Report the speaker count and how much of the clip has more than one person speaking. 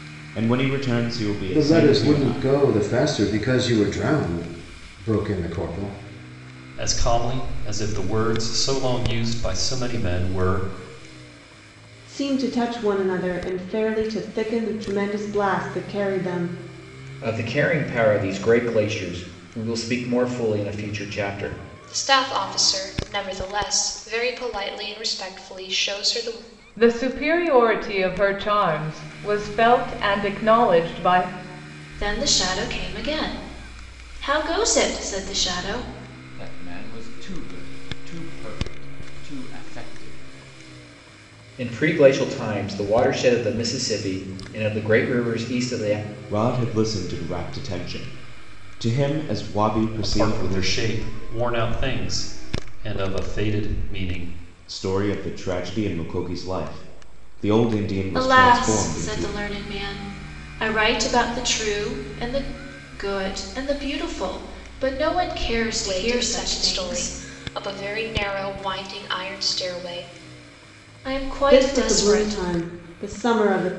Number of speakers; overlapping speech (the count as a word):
nine, about 7%